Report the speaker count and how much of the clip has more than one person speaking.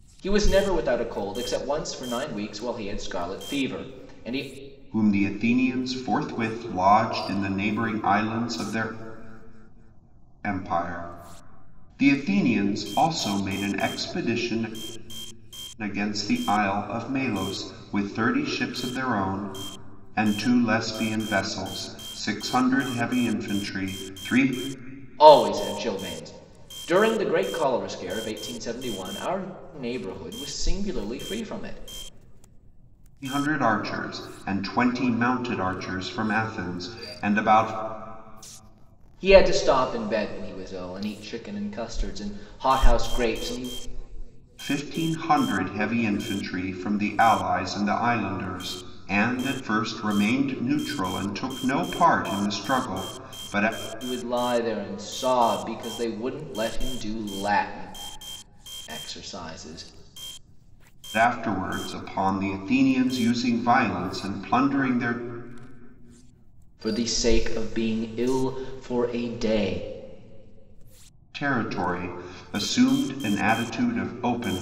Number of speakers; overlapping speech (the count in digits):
2, no overlap